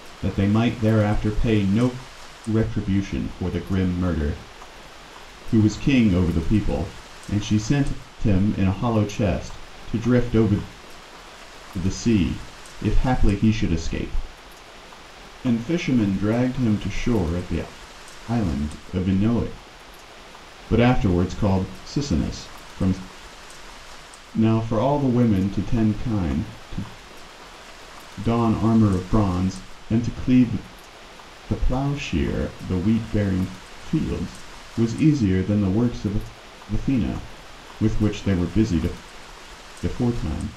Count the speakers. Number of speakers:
1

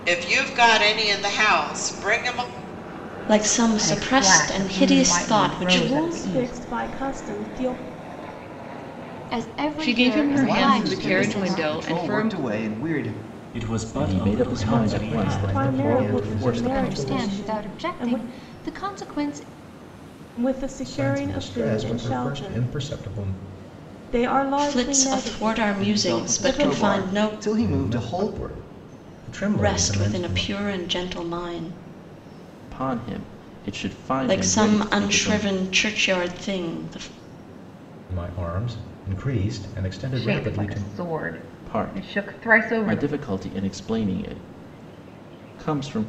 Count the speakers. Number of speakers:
10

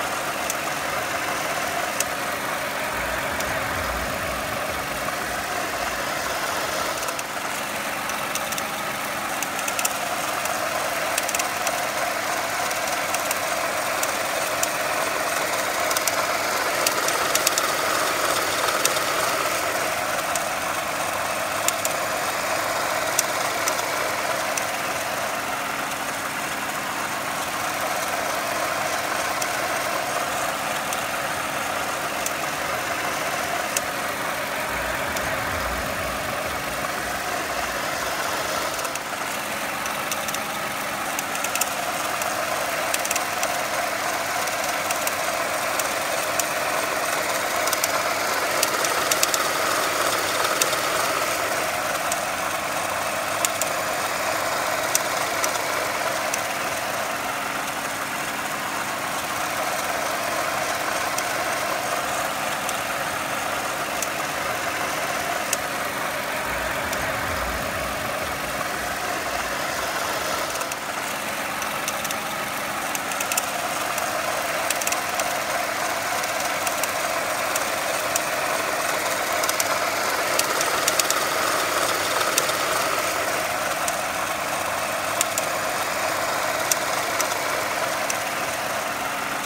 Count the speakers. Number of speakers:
0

